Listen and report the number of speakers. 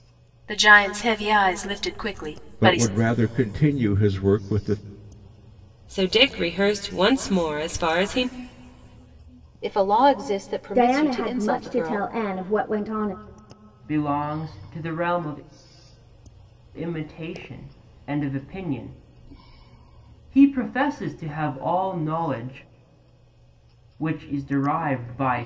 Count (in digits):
6